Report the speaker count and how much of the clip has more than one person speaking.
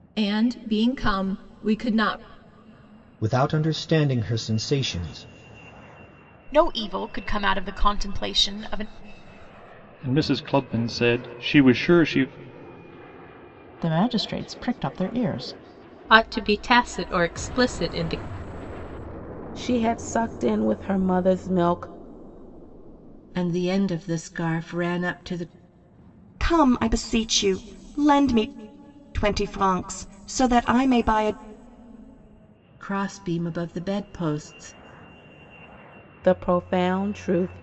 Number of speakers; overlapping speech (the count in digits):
9, no overlap